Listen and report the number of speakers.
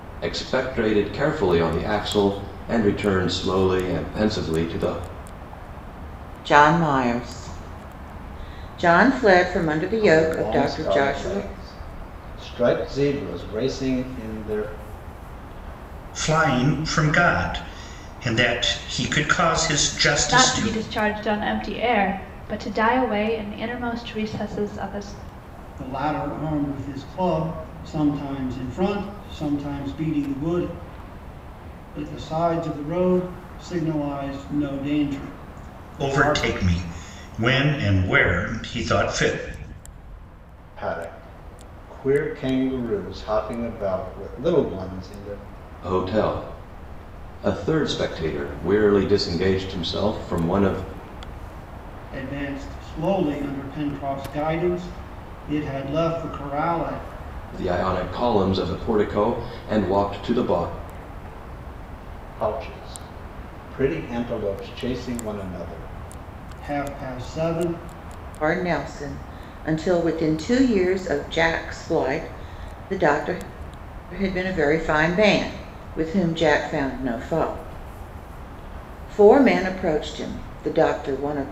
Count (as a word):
six